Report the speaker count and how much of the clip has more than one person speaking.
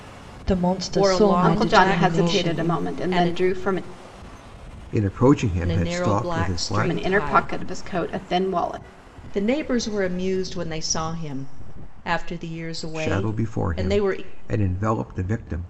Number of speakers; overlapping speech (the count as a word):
four, about 36%